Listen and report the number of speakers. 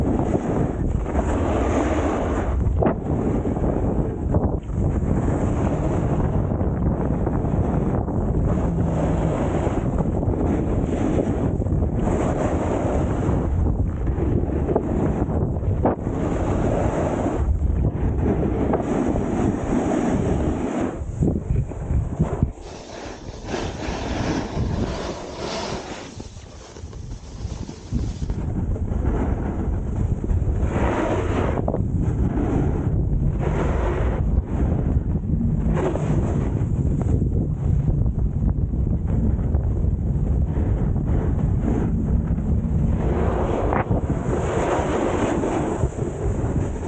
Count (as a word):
zero